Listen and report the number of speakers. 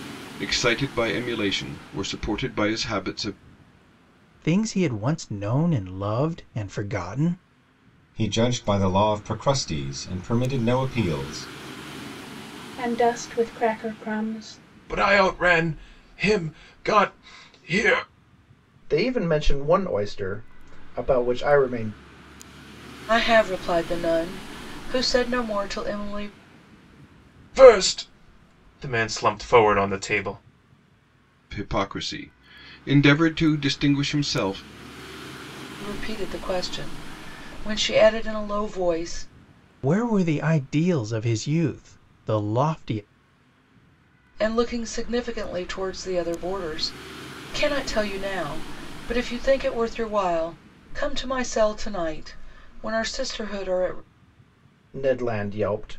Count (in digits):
7